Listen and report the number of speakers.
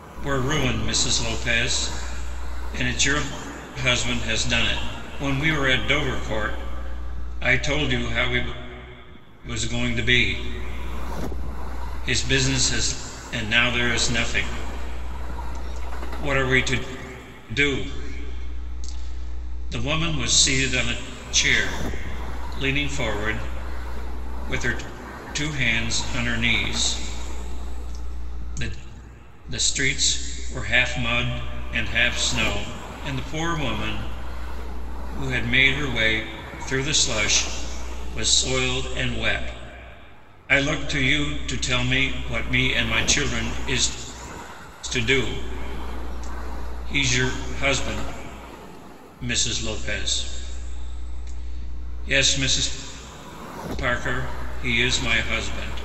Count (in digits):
1